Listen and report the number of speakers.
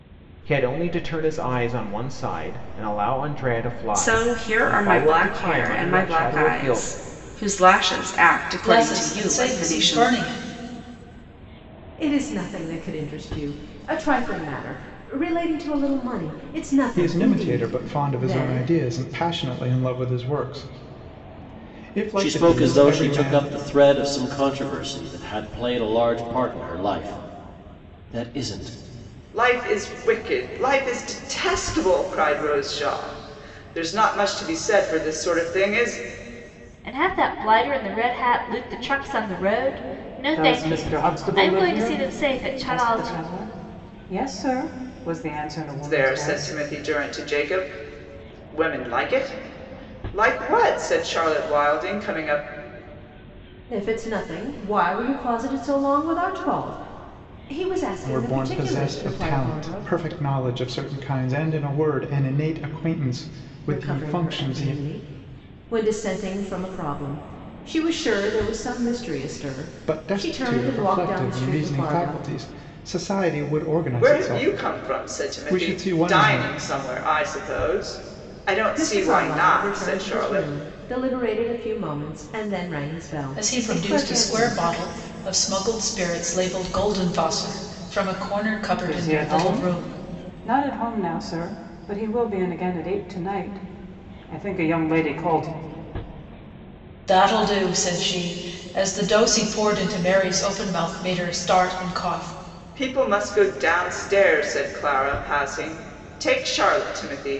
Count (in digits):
9